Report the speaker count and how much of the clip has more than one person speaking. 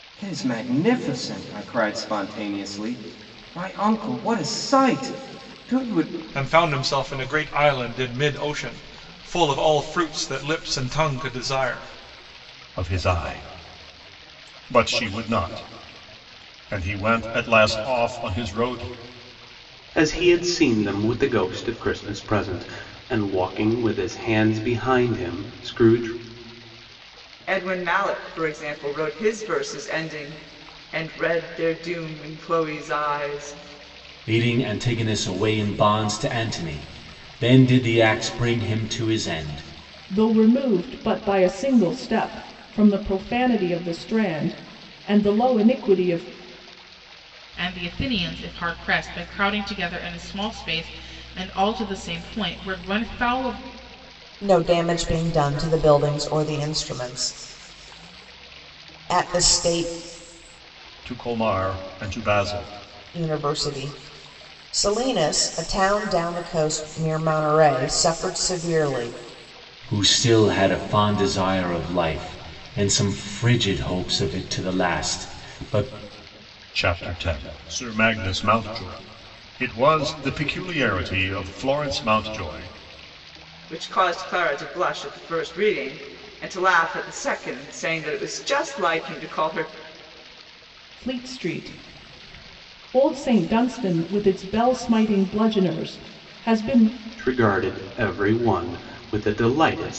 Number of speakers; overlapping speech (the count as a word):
nine, no overlap